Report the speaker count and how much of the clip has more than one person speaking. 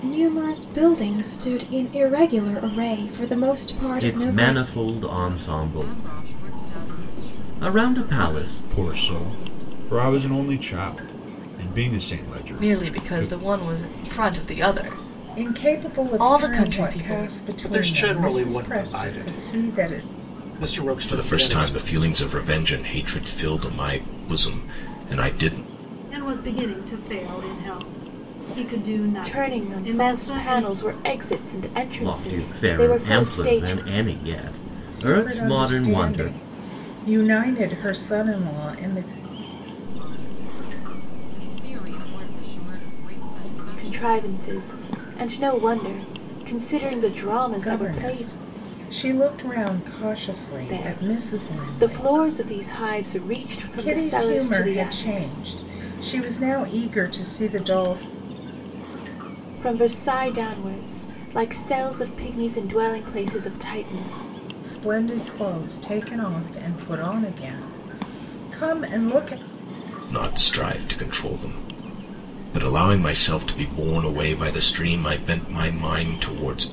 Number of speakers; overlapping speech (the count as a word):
ten, about 28%